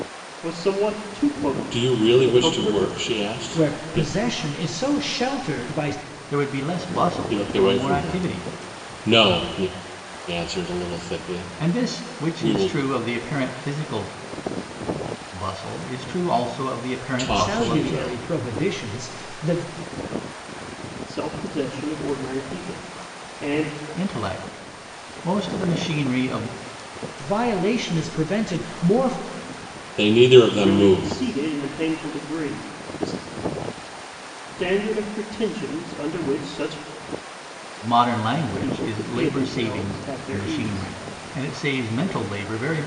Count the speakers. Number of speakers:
four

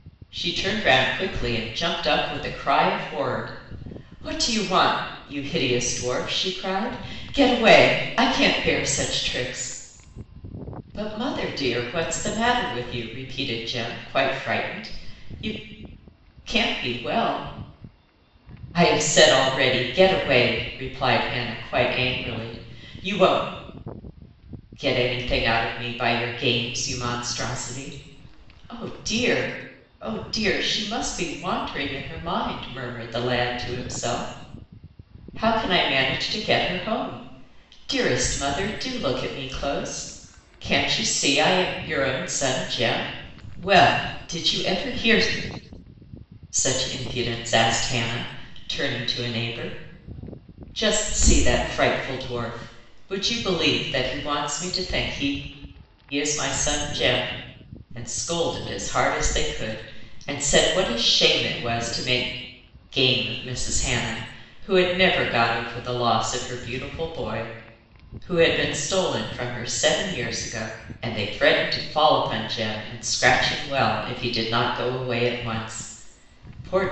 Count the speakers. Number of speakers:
one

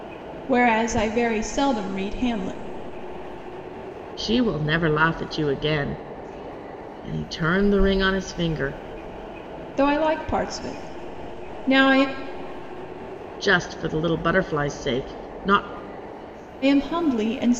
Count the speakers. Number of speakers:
two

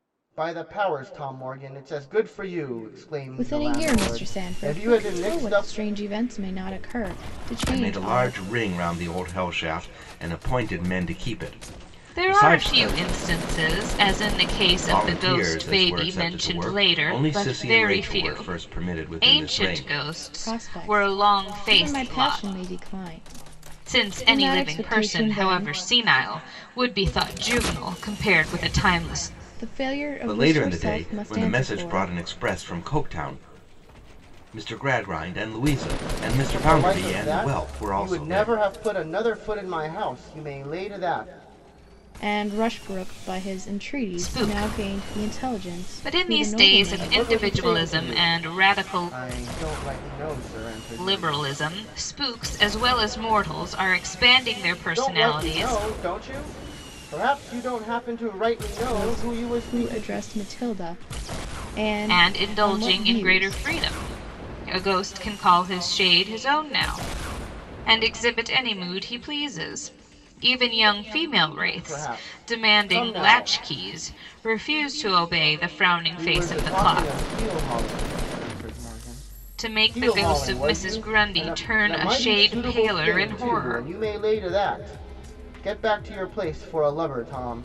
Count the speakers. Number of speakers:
four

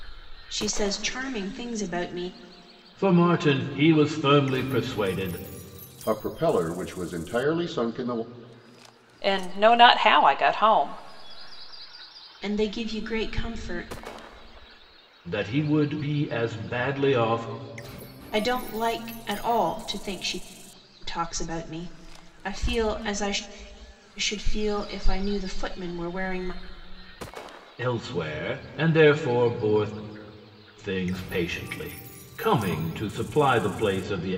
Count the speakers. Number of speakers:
four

